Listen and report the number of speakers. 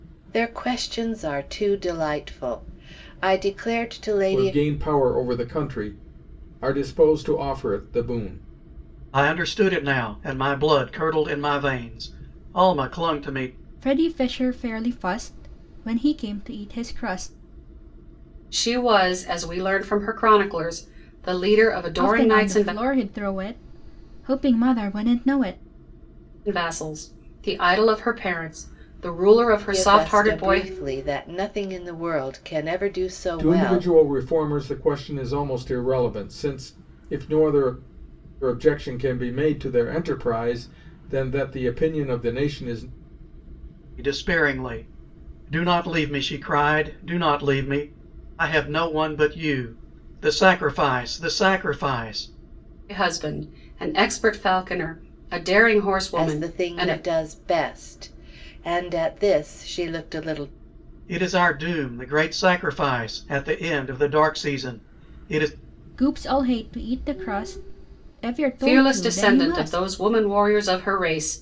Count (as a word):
five